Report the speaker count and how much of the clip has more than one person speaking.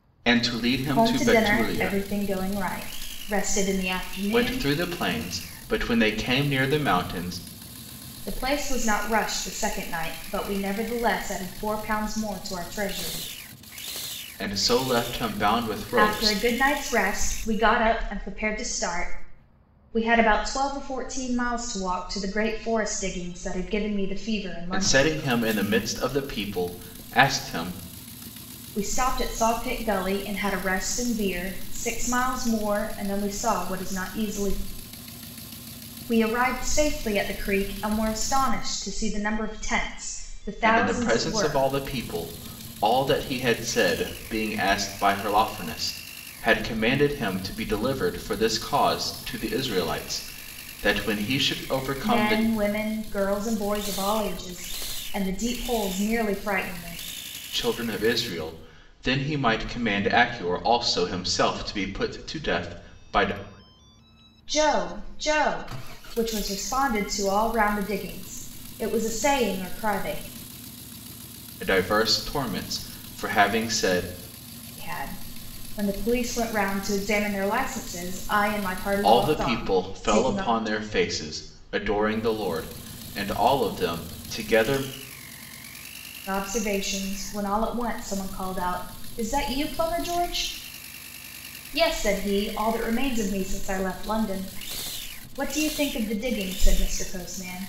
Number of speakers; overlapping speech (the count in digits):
2, about 6%